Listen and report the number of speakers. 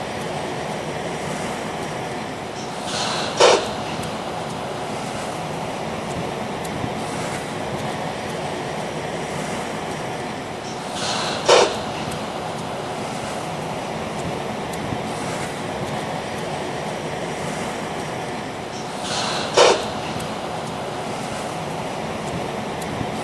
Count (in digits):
0